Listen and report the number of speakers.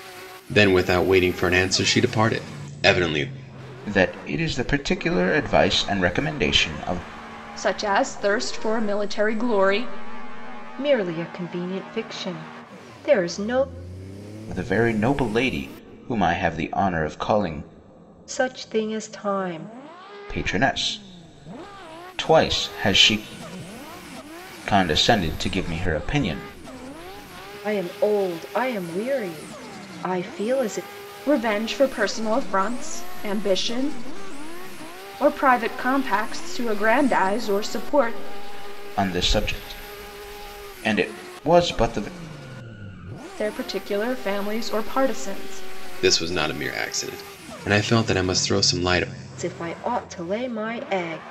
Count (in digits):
4